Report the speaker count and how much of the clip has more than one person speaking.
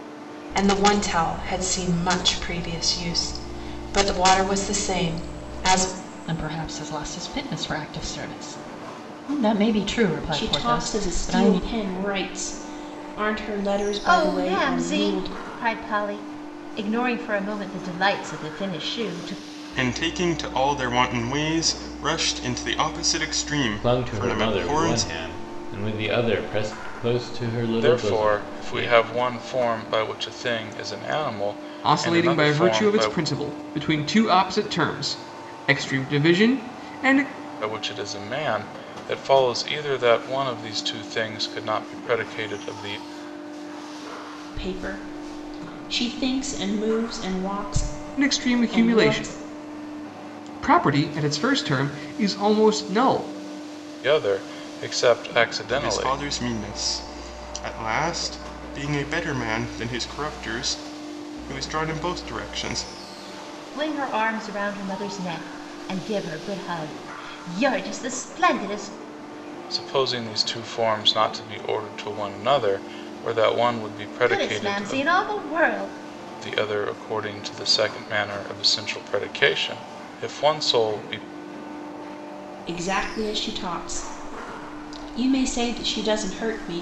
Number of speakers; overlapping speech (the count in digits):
8, about 11%